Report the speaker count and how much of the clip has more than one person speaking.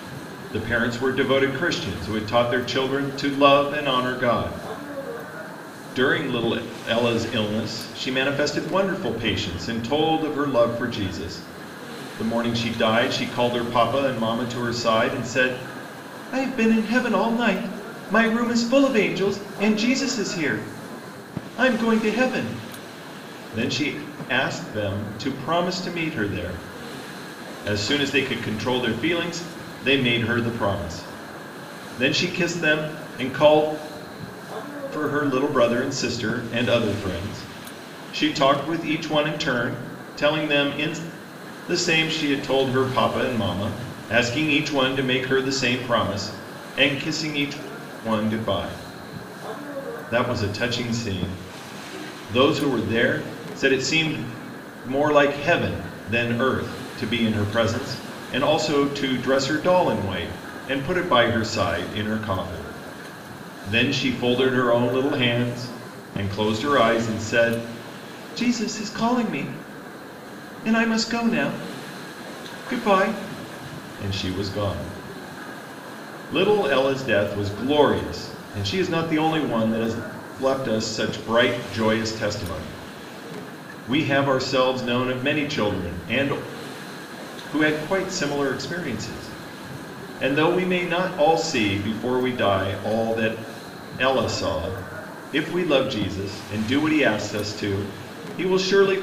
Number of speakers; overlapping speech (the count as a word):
one, no overlap